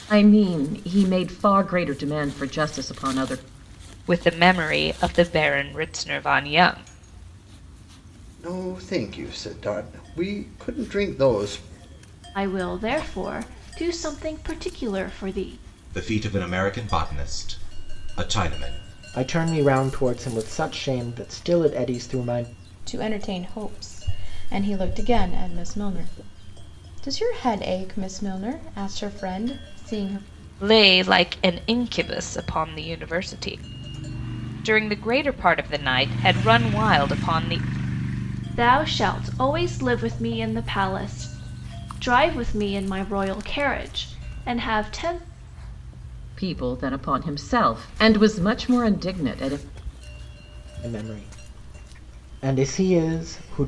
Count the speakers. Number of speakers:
7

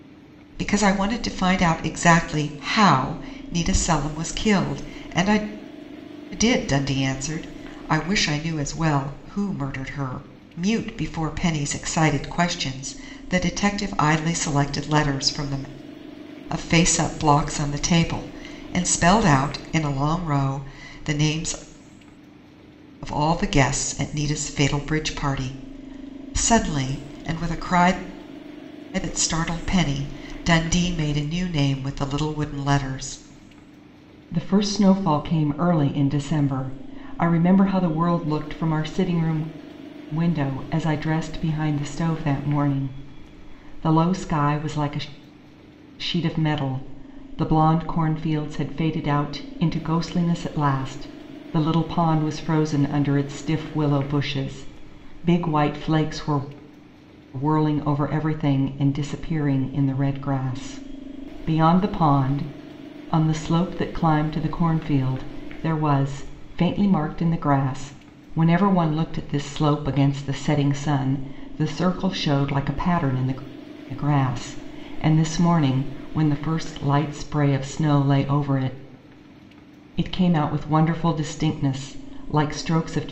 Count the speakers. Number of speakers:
1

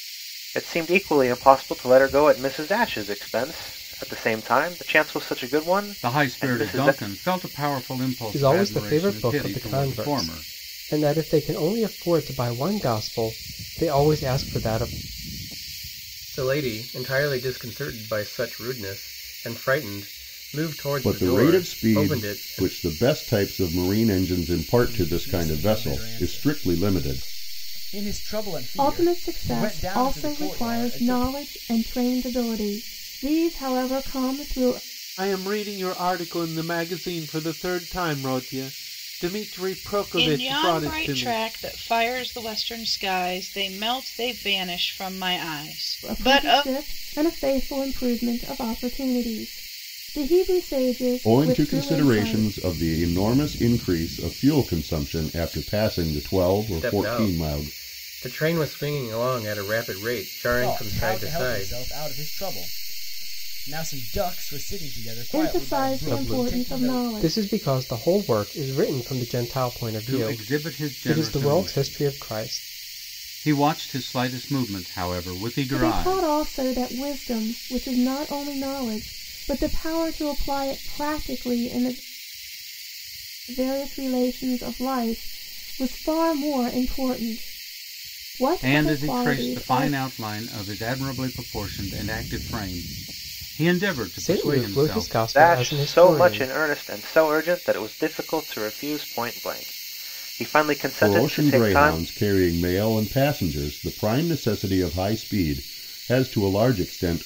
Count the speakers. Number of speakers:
9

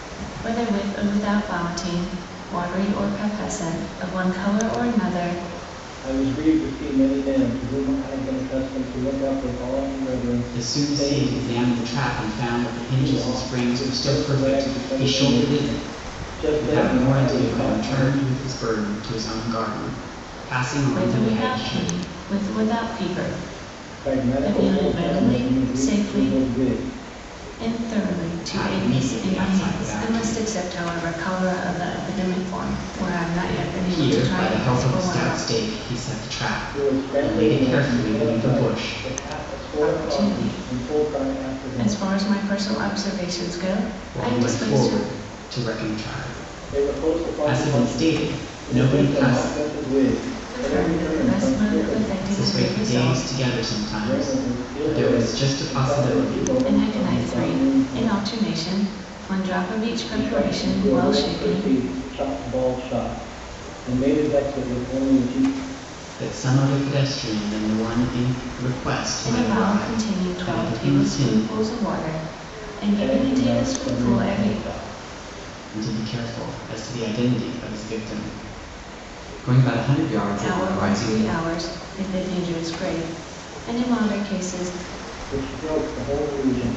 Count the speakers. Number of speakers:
3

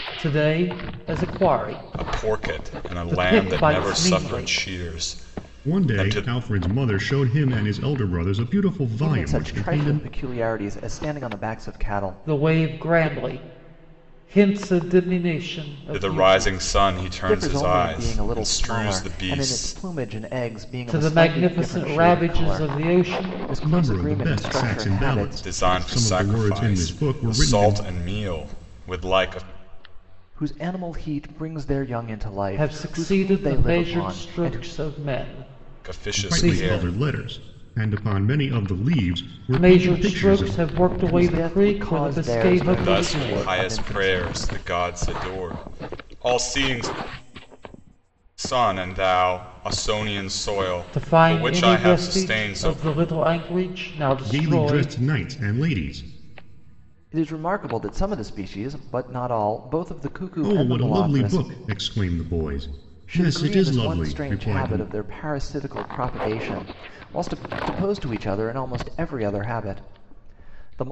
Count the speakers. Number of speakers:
4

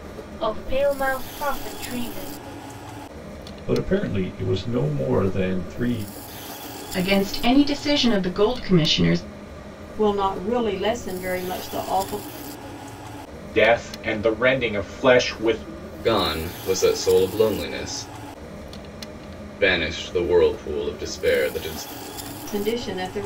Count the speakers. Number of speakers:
6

